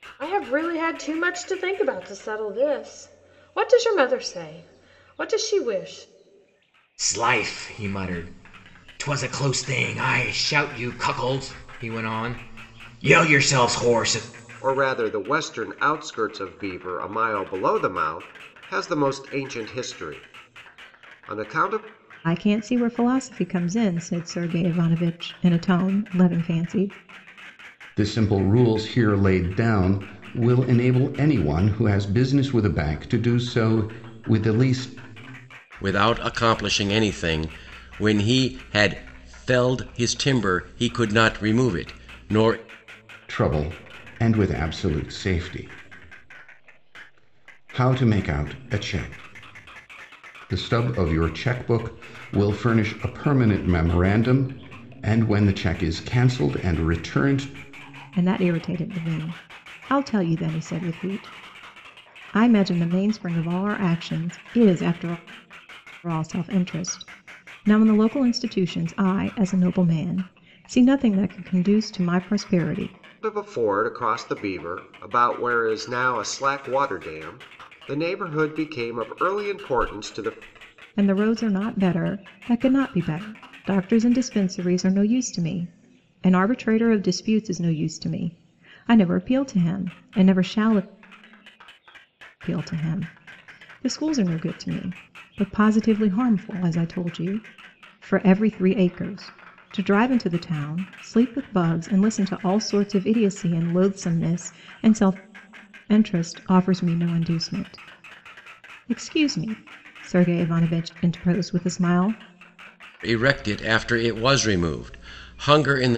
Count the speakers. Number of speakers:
6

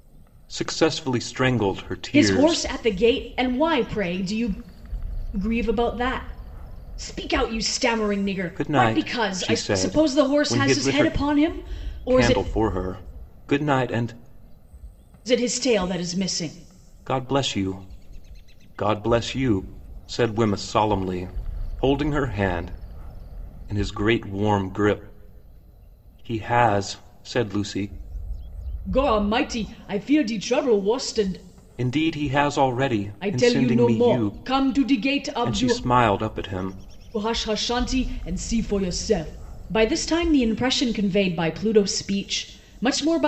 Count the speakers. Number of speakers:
2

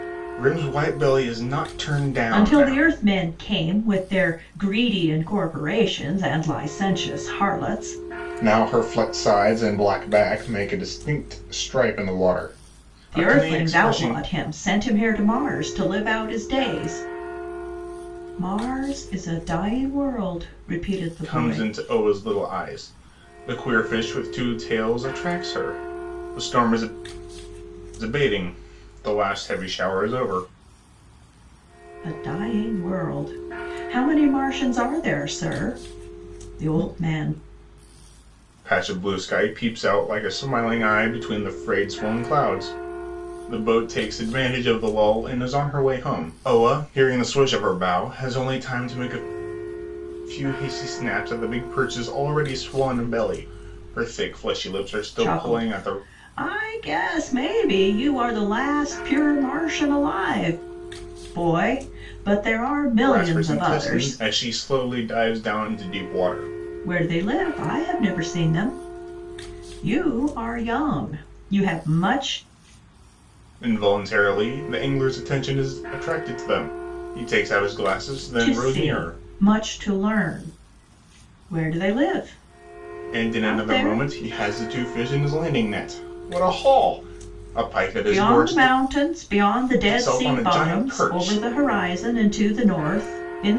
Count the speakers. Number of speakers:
2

